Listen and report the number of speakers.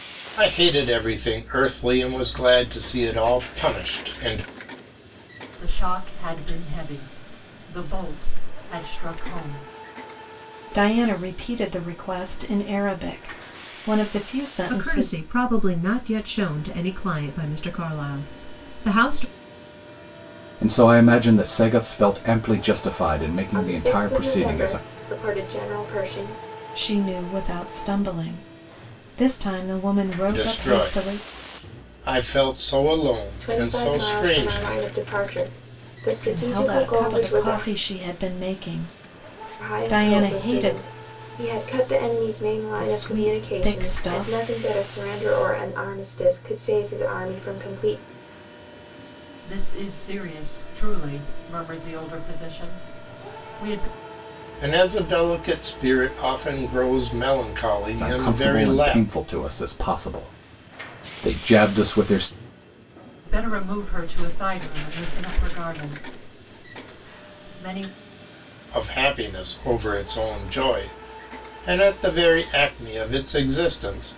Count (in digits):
6